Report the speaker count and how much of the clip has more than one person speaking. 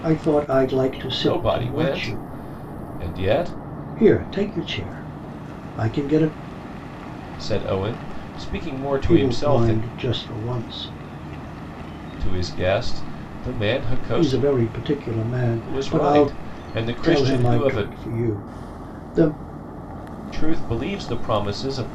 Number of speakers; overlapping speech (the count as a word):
two, about 18%